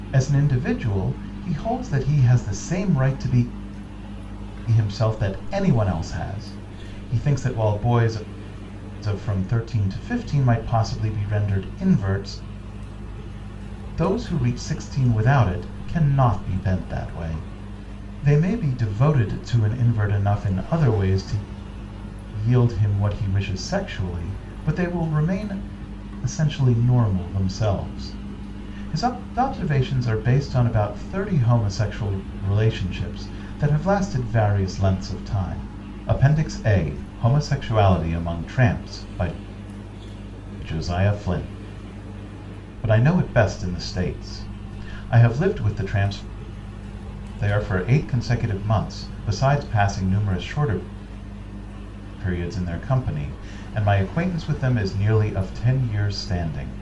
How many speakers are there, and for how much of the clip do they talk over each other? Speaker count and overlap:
one, no overlap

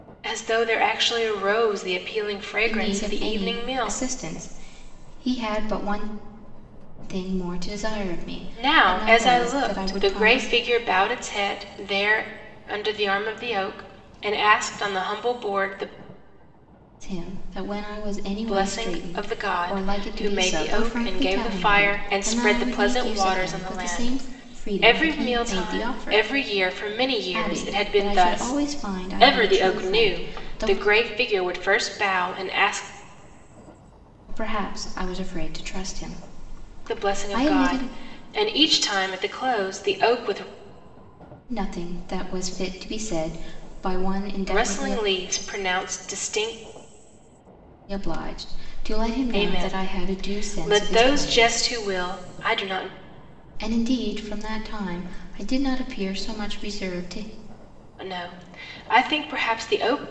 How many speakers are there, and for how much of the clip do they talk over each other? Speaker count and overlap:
two, about 30%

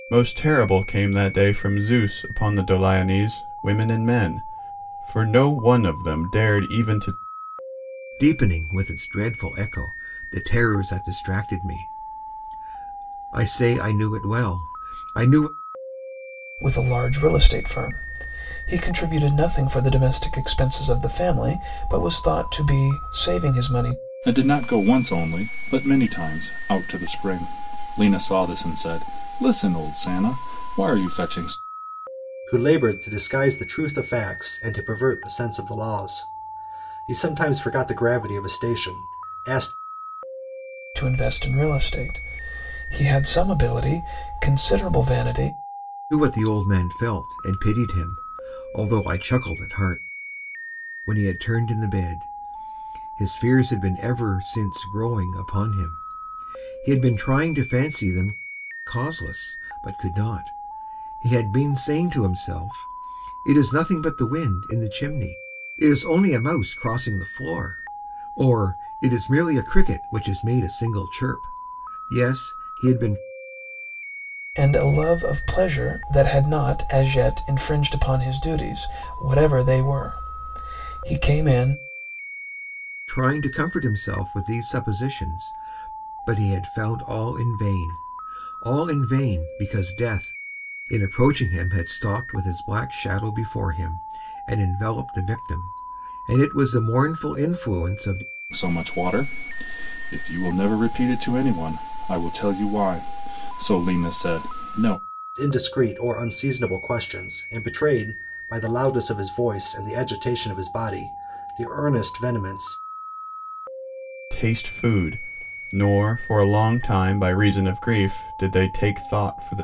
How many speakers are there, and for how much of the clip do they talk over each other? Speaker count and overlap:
five, no overlap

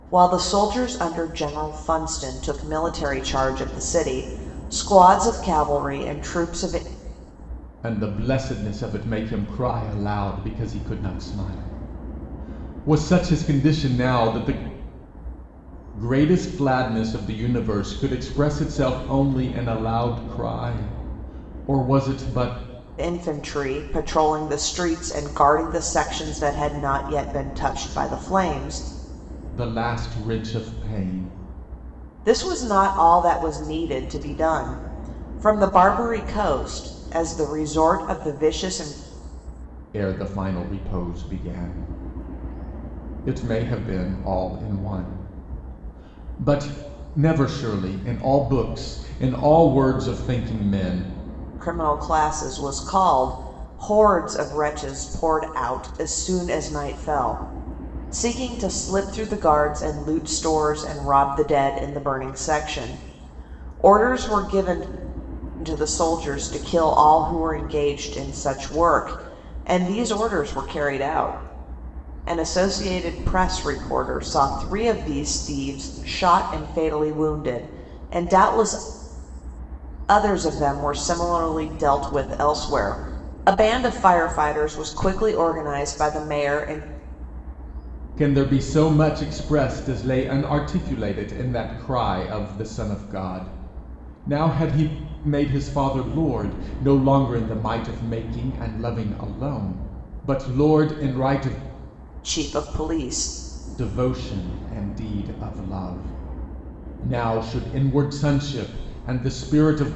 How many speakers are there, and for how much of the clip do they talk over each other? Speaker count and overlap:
two, no overlap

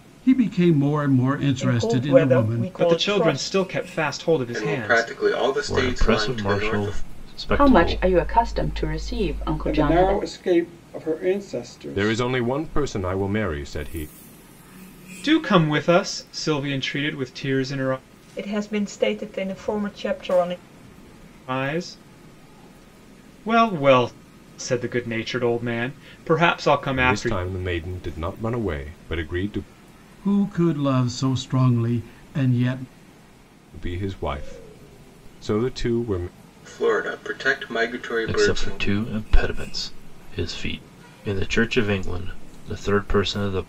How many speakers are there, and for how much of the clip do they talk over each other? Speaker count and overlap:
eight, about 15%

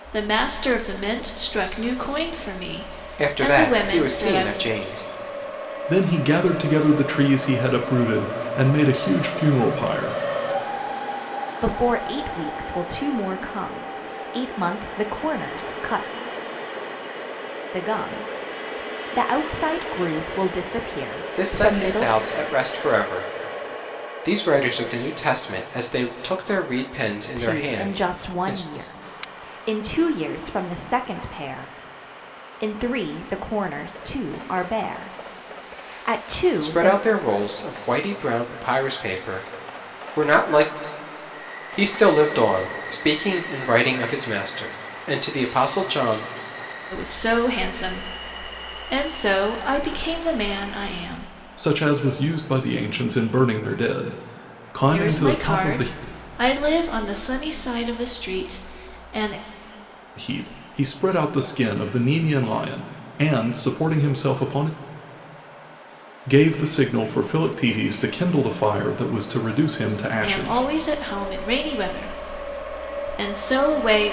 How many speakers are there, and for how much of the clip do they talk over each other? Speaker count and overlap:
four, about 7%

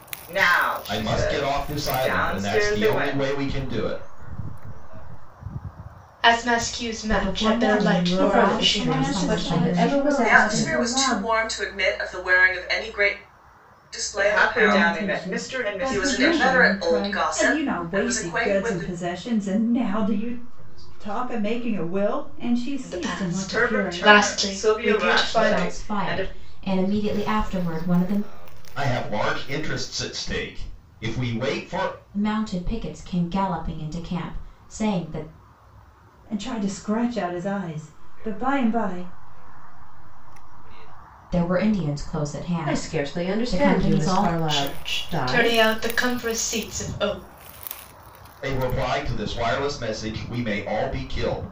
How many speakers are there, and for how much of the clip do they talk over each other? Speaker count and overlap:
eight, about 50%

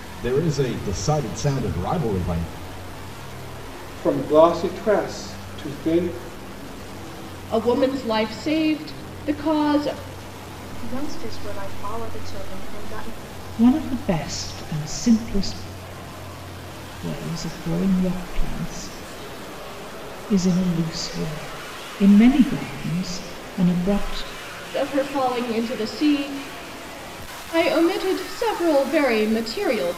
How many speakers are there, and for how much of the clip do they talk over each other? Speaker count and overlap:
five, no overlap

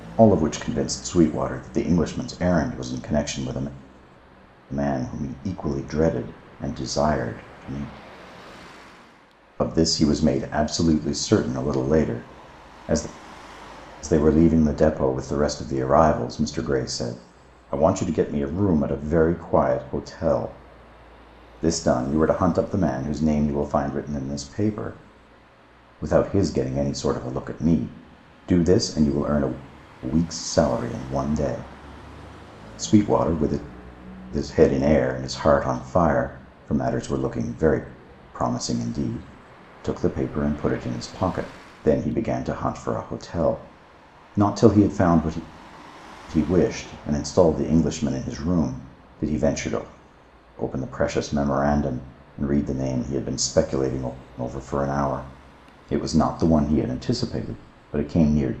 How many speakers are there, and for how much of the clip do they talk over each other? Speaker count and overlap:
one, no overlap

